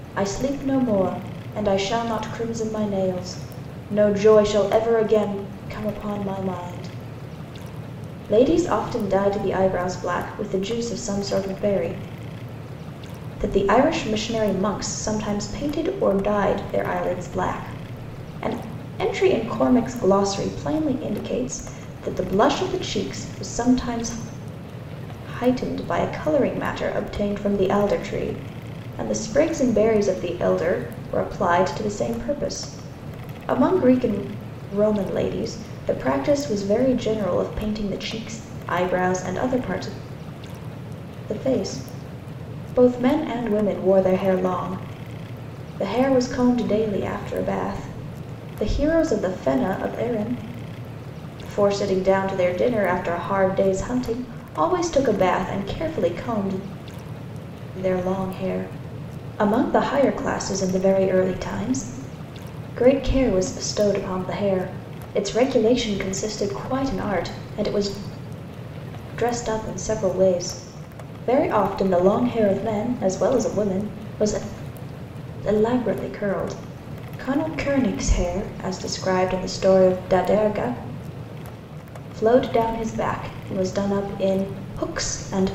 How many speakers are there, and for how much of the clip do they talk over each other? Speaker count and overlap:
1, no overlap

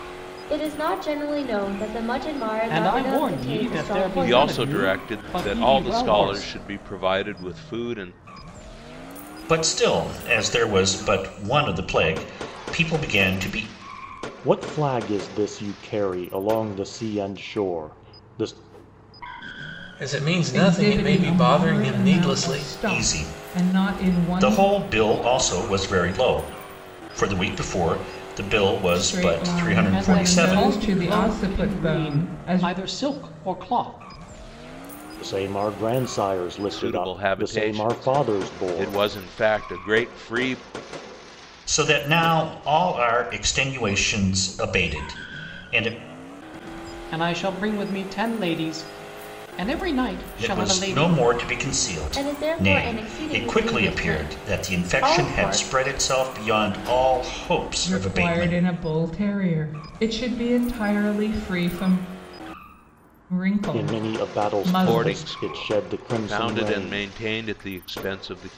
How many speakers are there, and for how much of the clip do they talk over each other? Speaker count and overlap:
7, about 33%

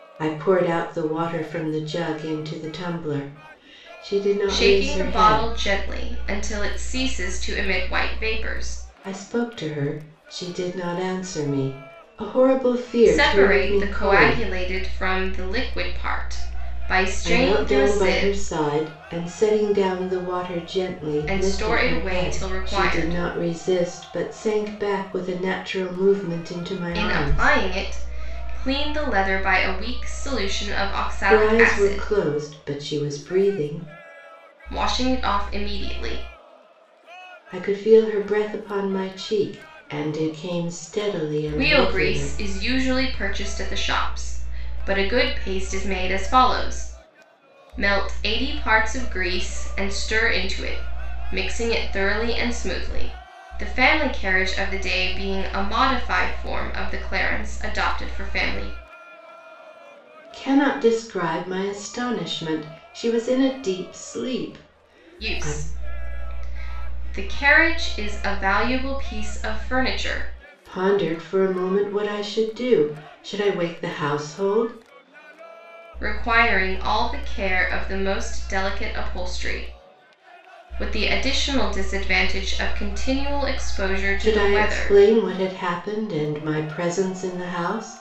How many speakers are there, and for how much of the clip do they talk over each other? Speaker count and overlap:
2, about 10%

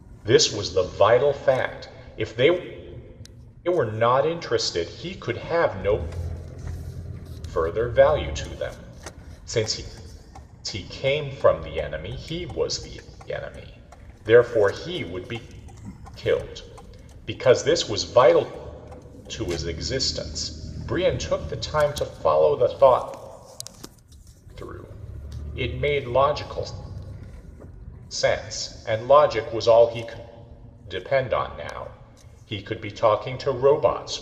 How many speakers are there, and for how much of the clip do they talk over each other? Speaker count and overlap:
1, no overlap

